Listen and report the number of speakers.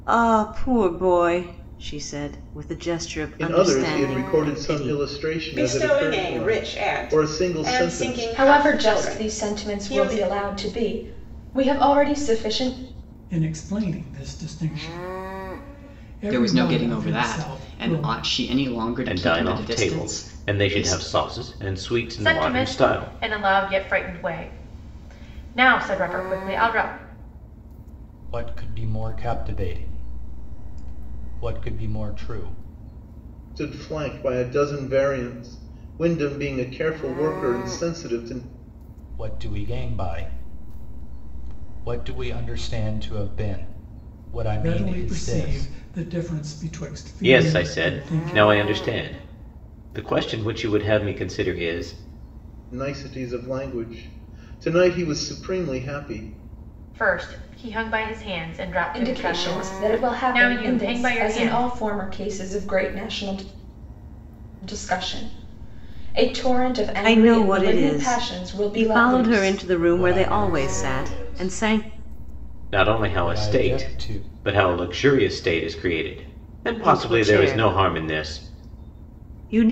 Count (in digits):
9